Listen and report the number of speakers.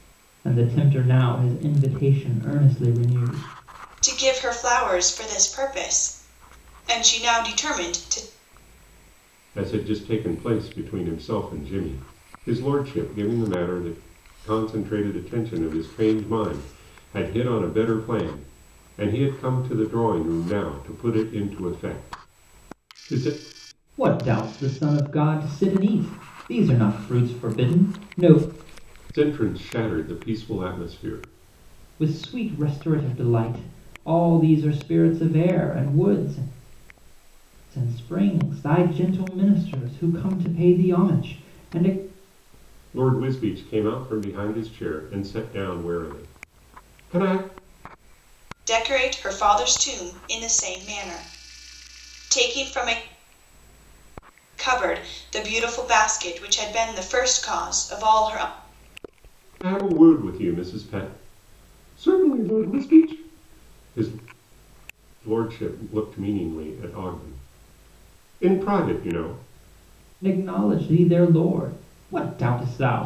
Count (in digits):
3